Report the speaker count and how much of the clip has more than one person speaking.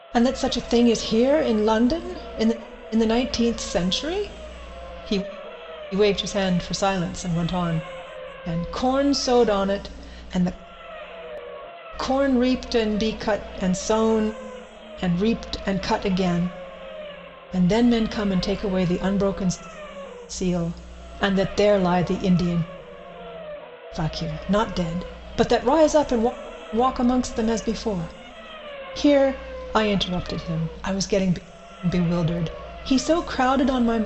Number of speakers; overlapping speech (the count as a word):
one, no overlap